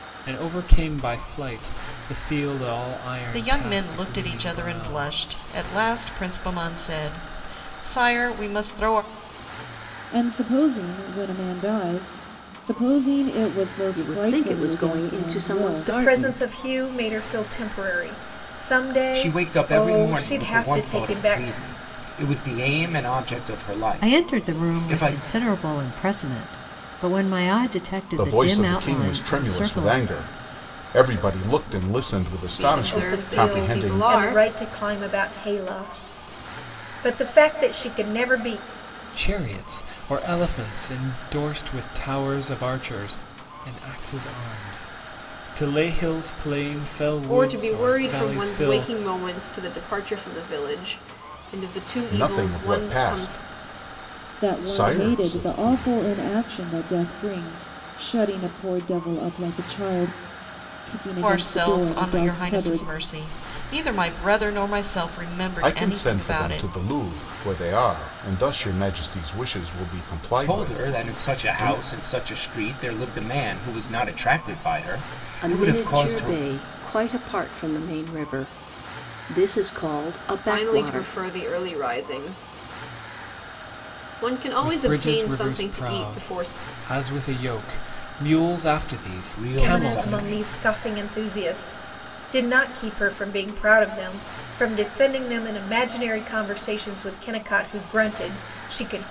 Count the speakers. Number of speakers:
nine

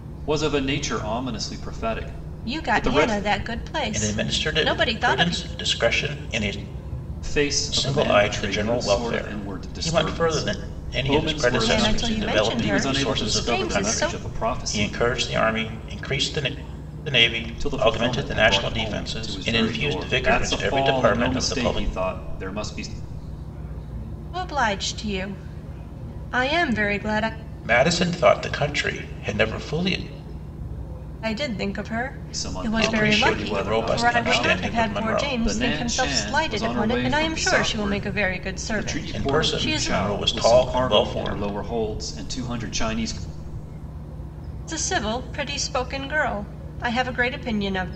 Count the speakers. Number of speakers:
three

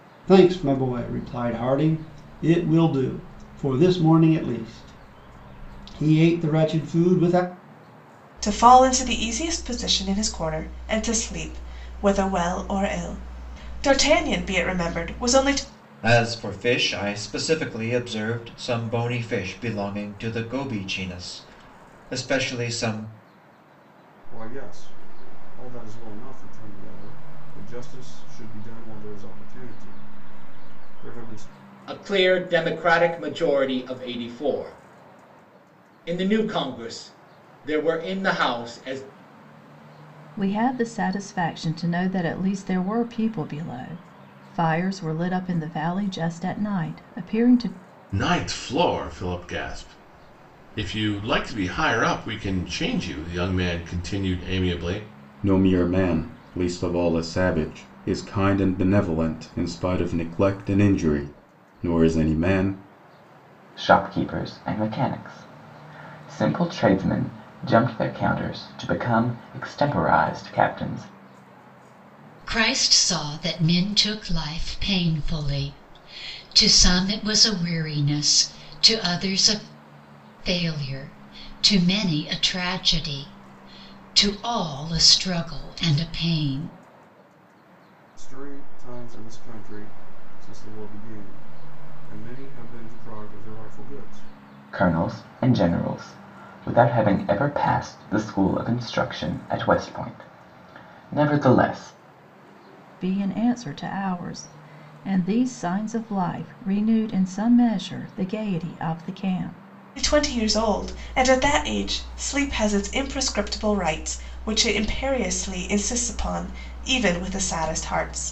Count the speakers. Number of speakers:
ten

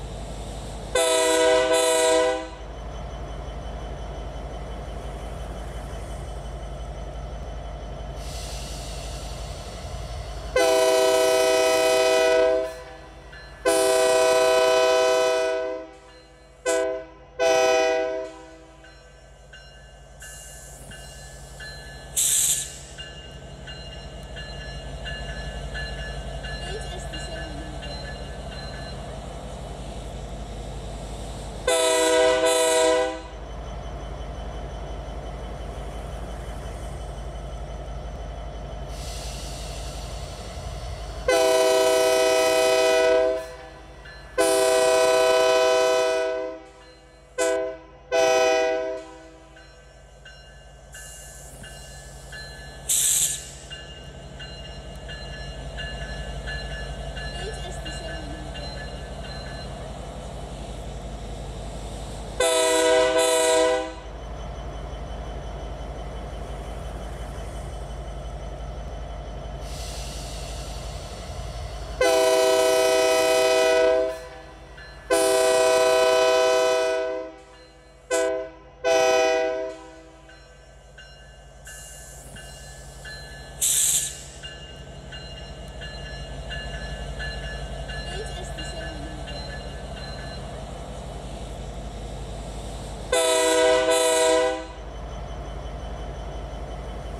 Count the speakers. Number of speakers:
zero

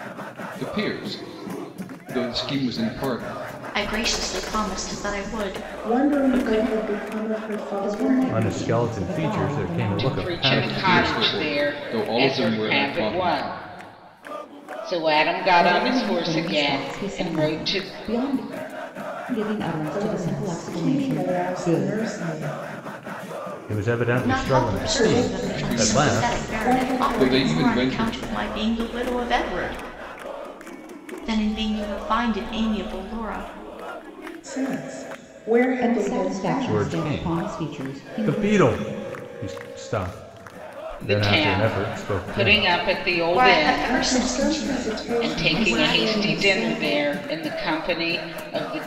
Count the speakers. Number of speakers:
six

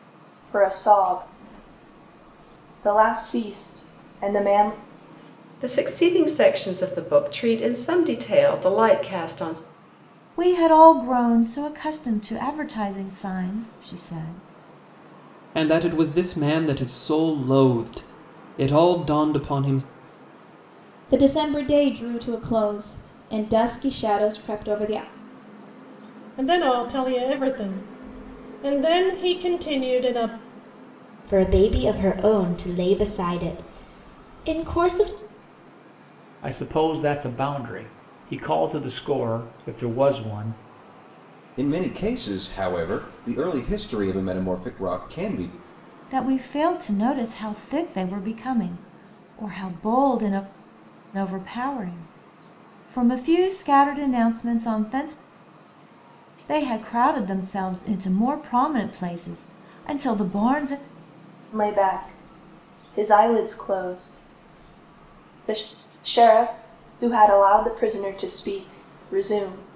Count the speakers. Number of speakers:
nine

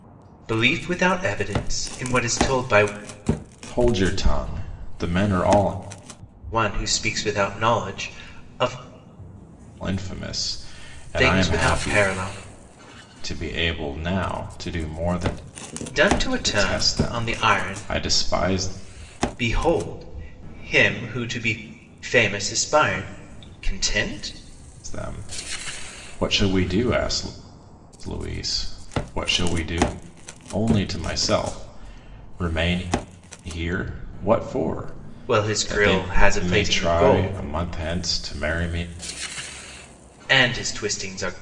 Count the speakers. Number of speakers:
two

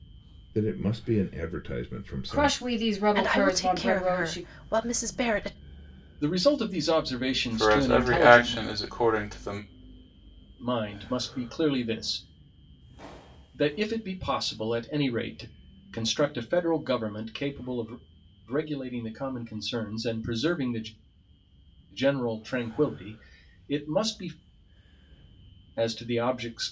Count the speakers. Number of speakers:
five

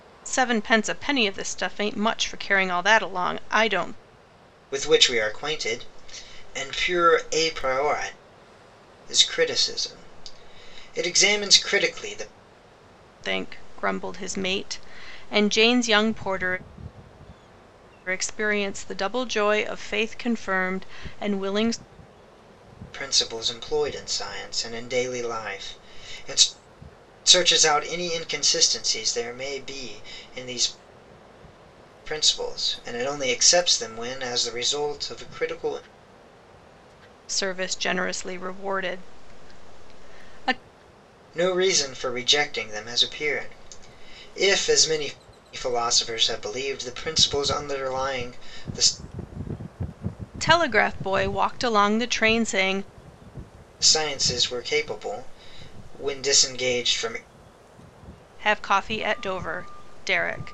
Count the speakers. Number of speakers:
two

